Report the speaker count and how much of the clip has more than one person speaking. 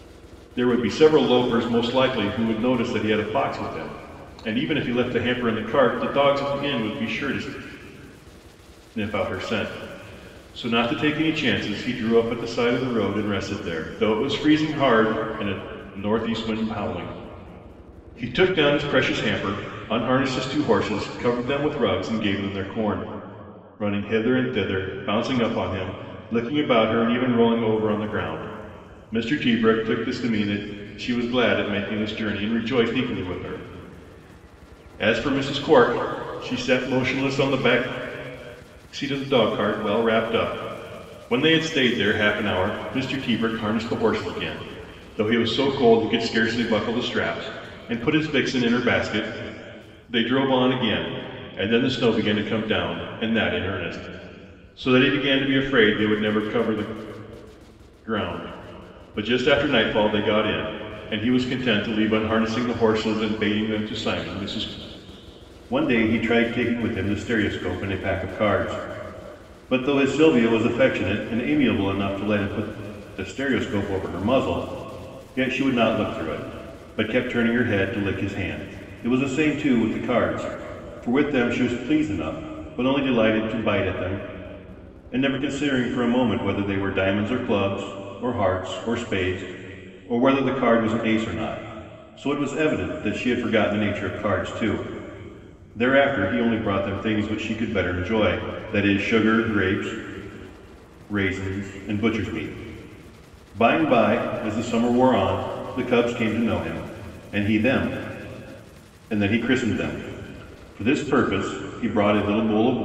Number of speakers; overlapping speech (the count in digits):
1, no overlap